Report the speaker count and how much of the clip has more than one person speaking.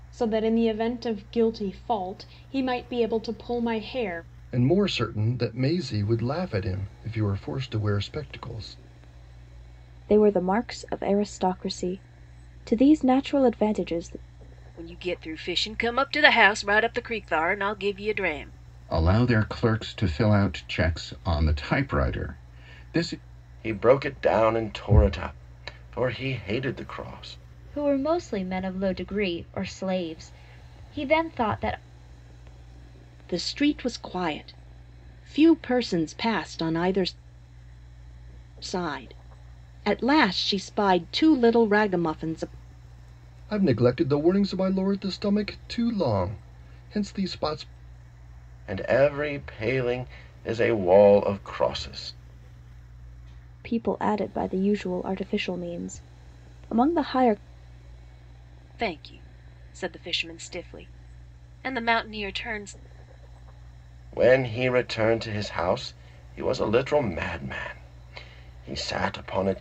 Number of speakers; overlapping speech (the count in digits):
8, no overlap